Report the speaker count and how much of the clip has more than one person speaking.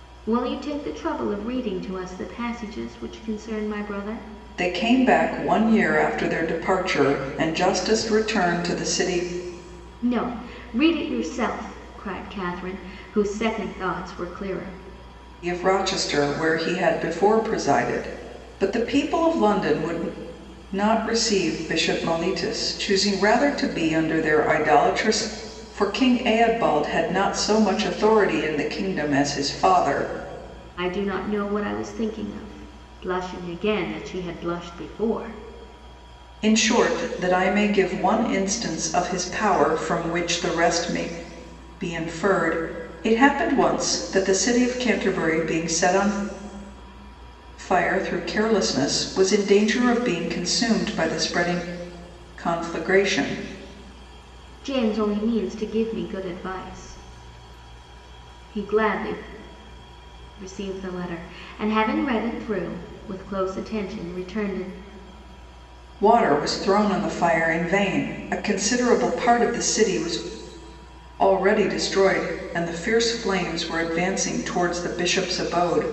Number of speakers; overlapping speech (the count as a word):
two, no overlap